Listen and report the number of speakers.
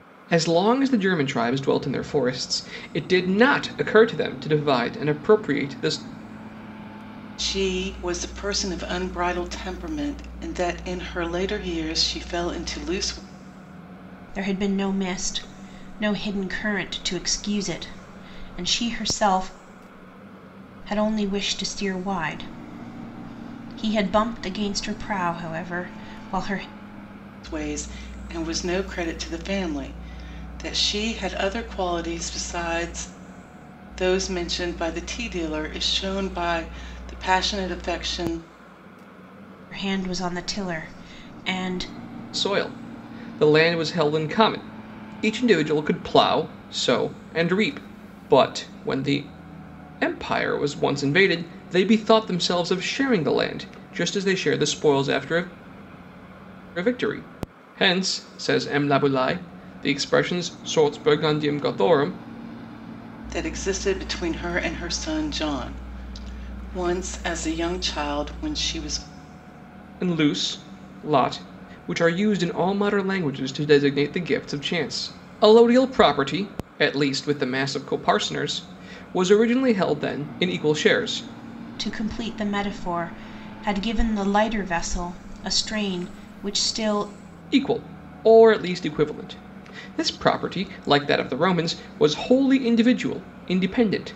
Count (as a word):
three